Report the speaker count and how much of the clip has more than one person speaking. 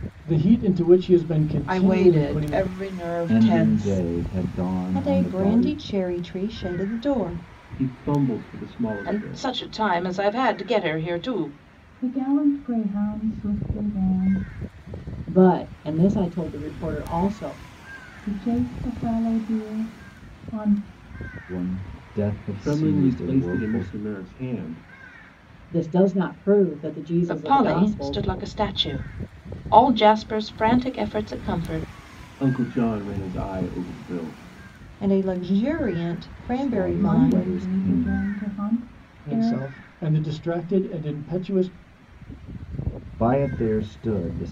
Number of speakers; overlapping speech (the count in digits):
8, about 17%